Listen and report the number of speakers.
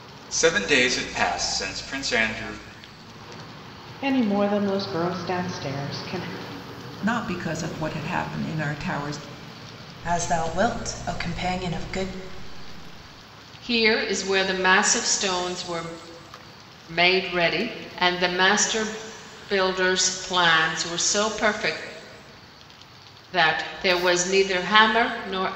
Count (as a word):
five